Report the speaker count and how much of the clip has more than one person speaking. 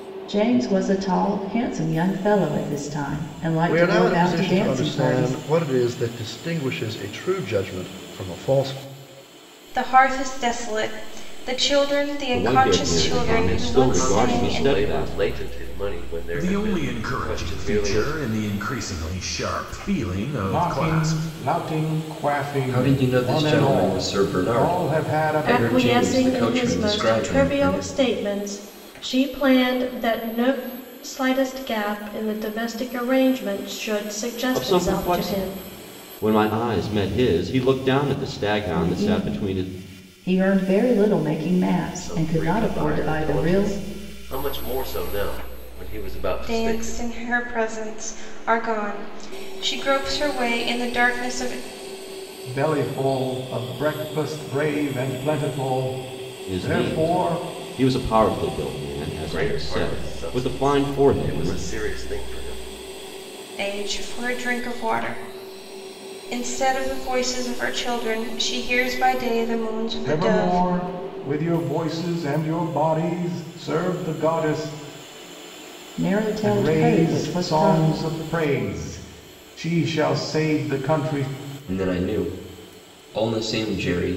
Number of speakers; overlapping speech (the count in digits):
9, about 27%